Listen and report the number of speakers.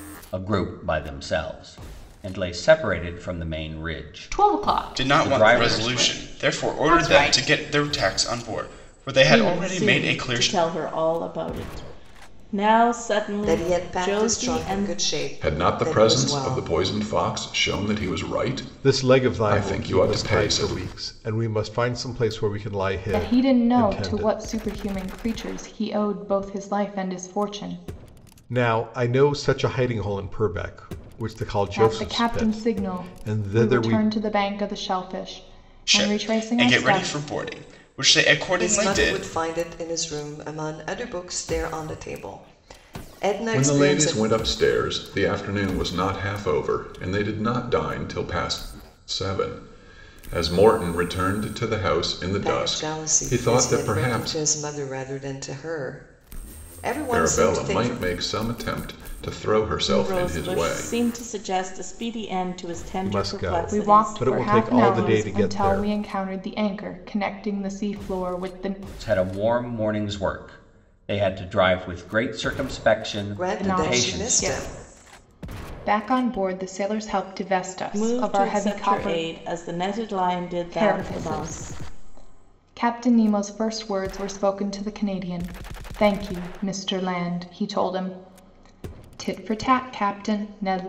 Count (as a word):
eight